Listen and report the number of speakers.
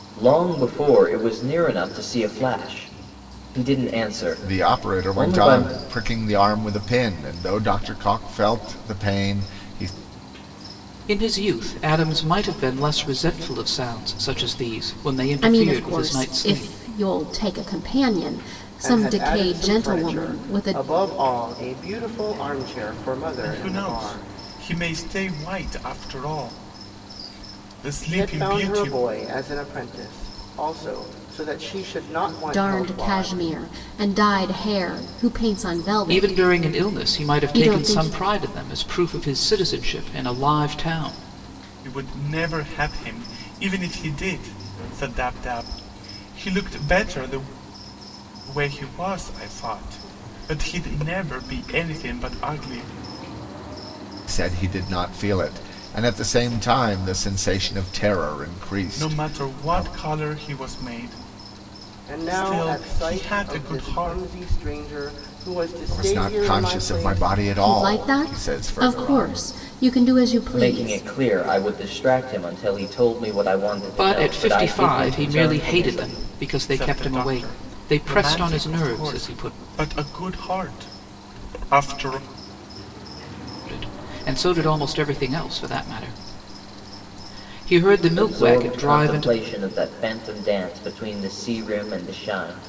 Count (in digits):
6